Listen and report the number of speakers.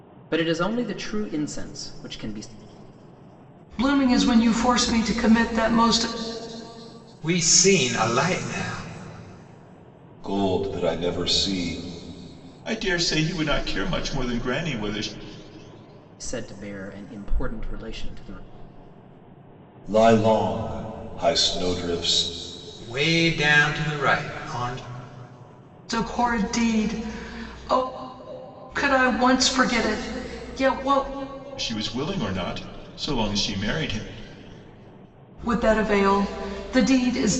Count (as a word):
five